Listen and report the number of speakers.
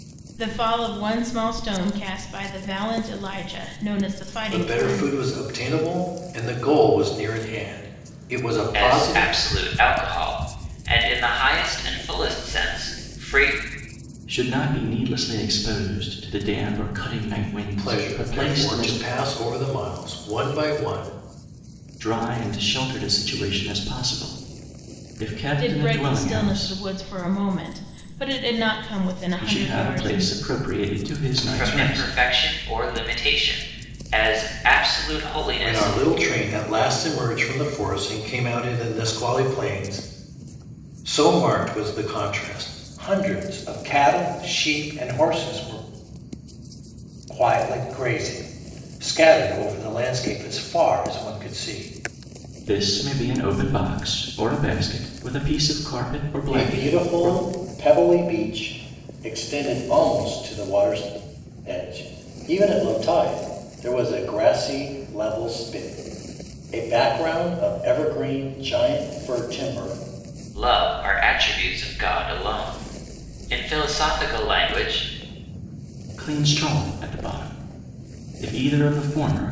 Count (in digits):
4